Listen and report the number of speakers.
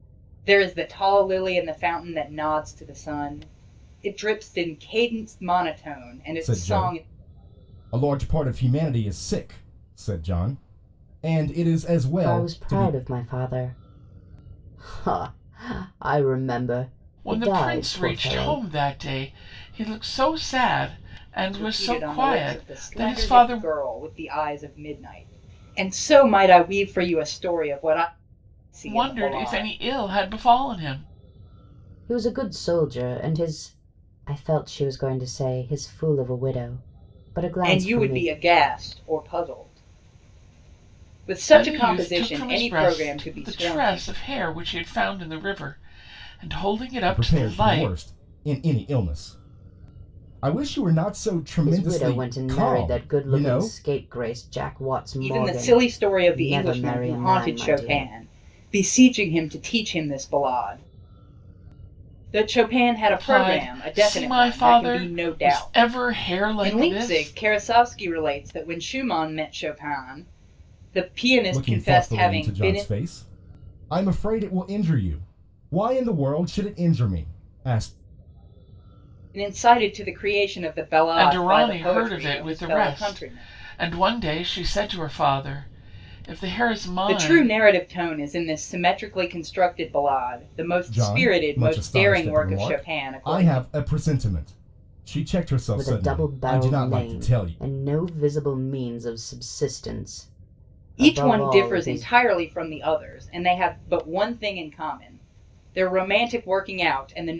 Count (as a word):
four